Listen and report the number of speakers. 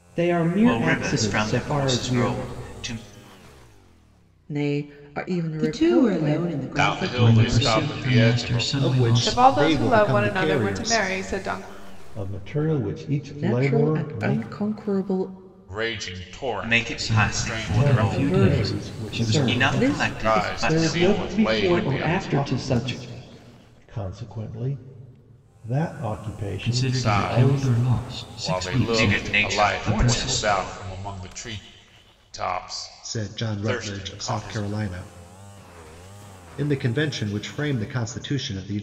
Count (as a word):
nine